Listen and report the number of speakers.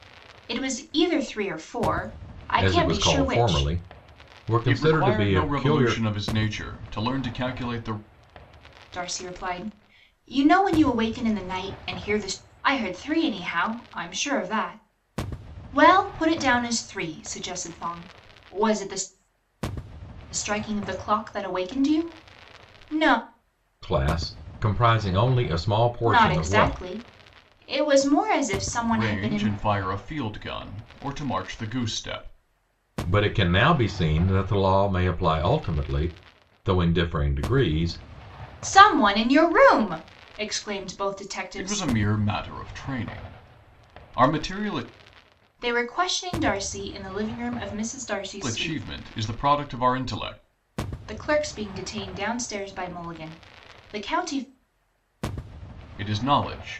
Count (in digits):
3